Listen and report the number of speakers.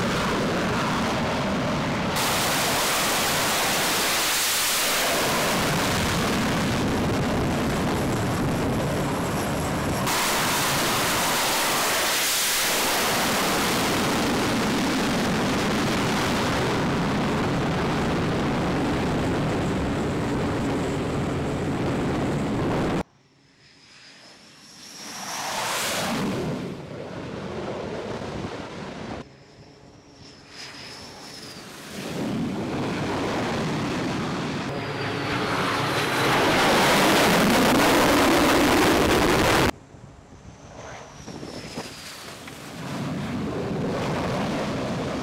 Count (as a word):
zero